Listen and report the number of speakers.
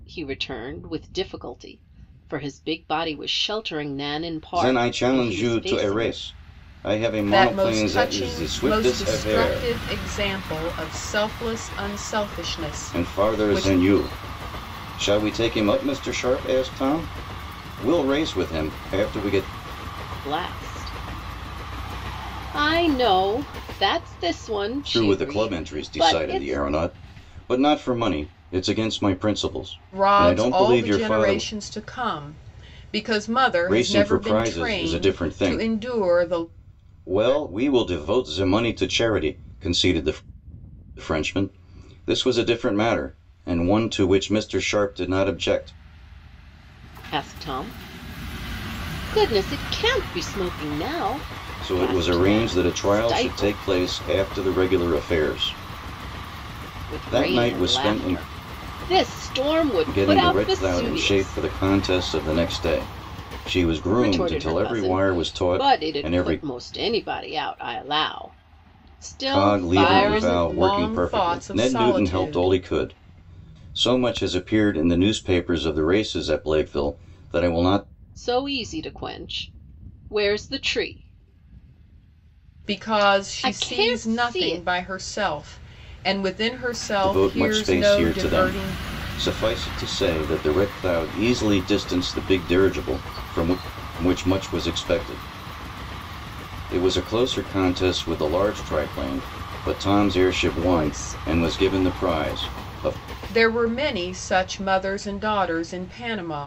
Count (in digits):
3